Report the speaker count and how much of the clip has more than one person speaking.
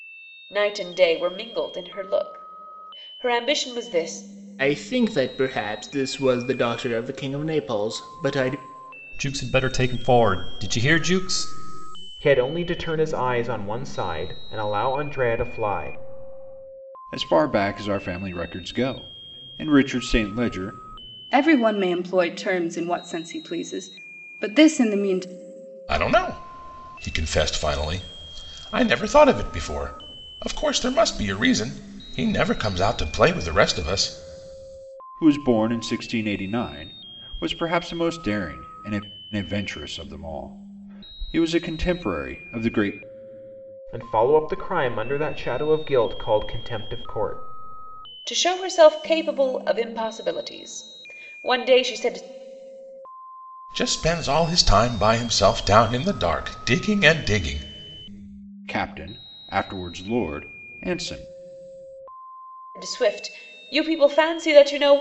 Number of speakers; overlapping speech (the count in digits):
7, no overlap